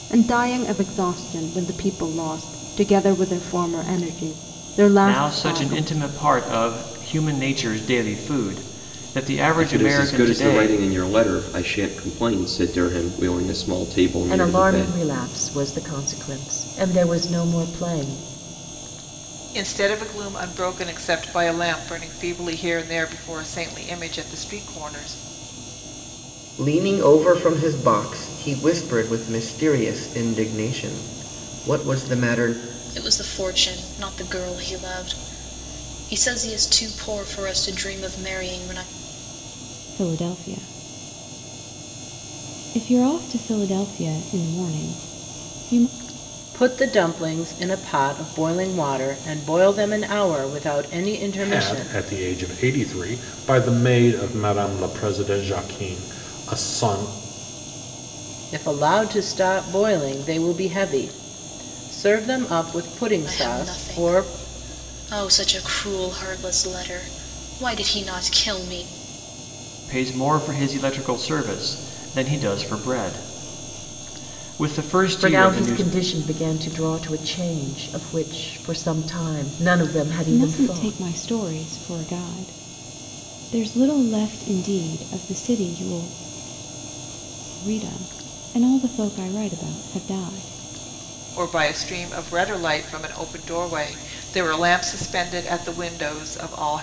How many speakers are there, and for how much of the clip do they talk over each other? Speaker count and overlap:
ten, about 6%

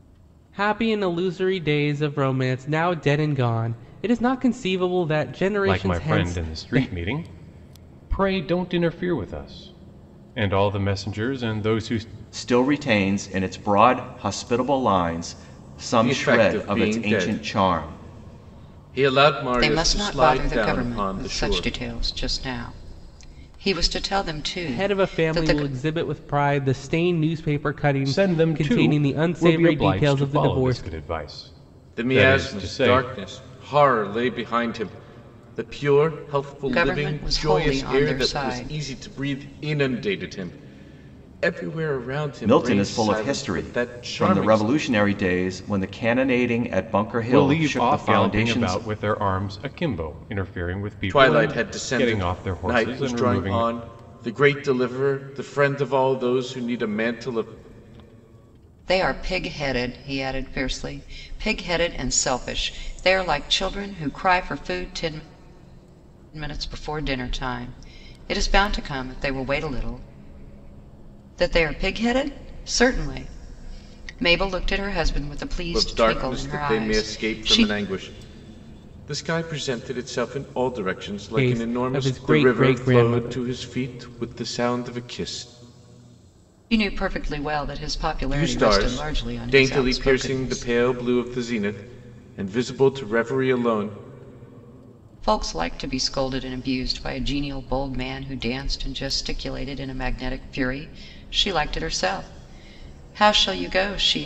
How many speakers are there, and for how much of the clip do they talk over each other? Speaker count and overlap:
five, about 25%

